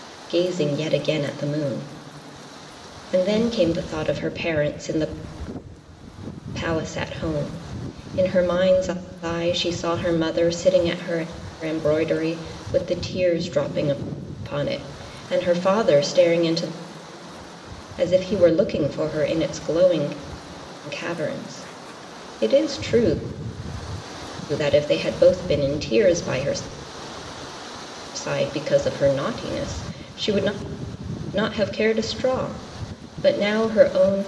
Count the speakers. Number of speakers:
one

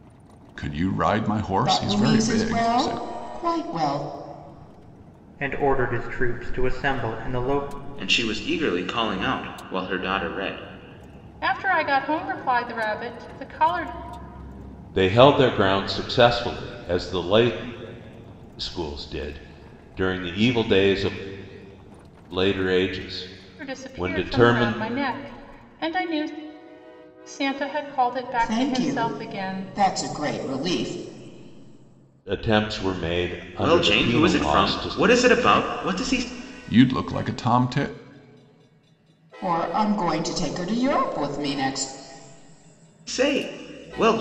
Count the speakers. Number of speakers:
six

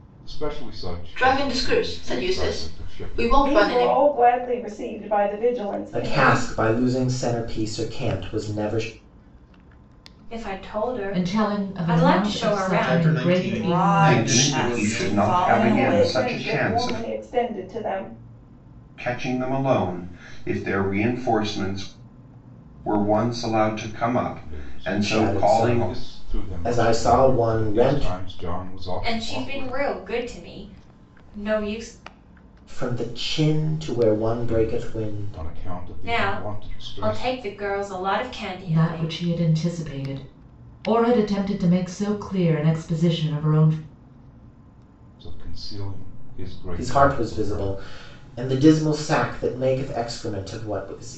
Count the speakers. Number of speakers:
nine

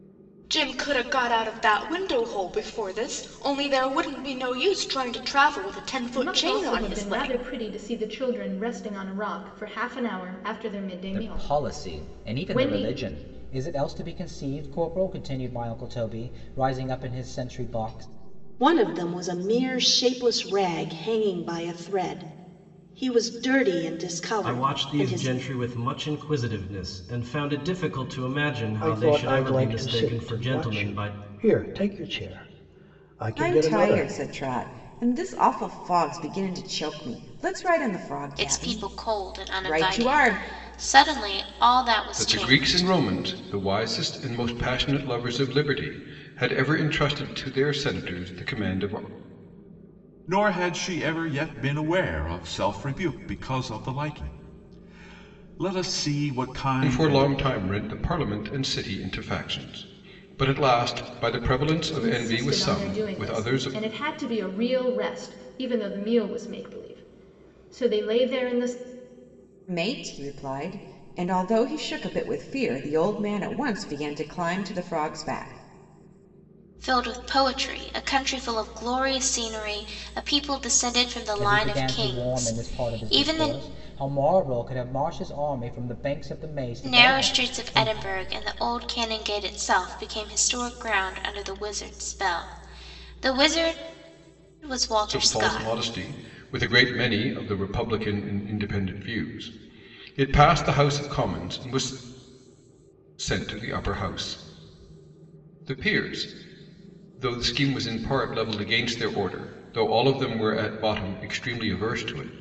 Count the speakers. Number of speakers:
ten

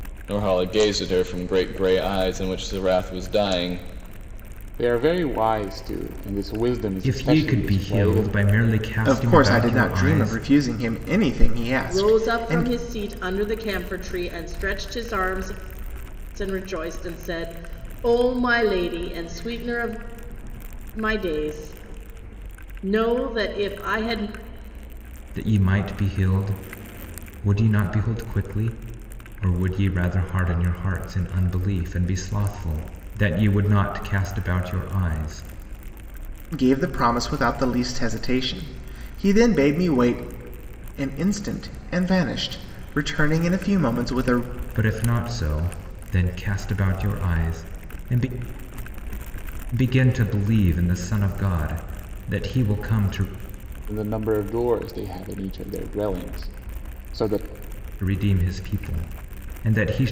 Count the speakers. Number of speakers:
five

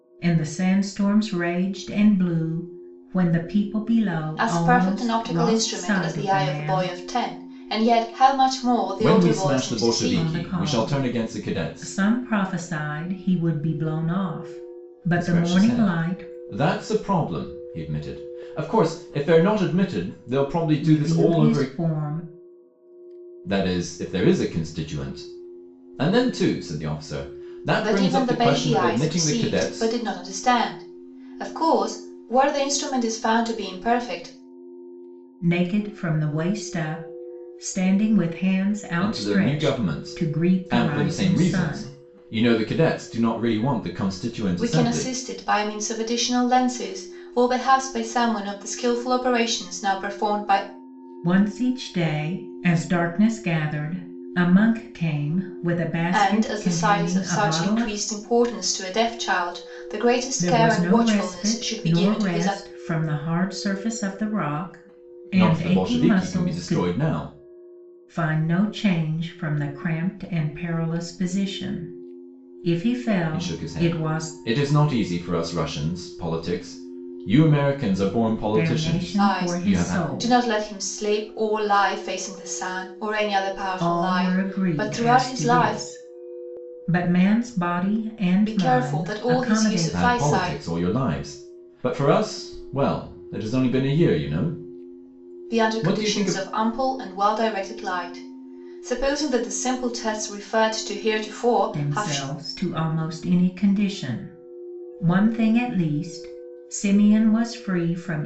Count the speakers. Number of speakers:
three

